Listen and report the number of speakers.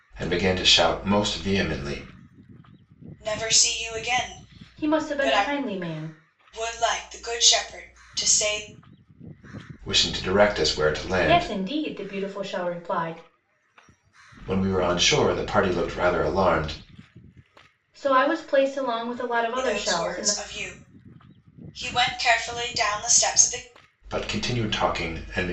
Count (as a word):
three